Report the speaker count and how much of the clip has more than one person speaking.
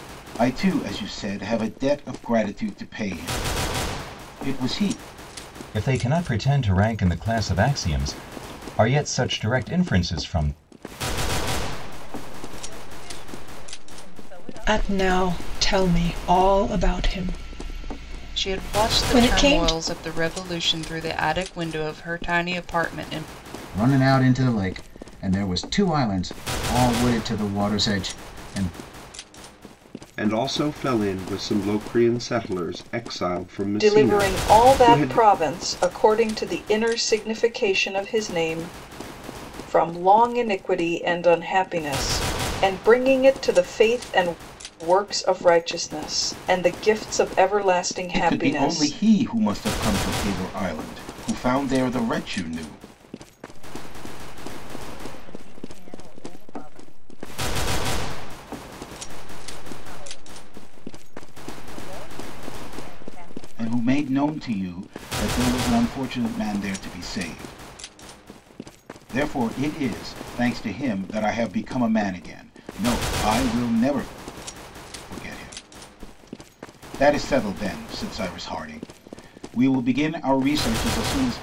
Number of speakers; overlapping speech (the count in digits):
8, about 7%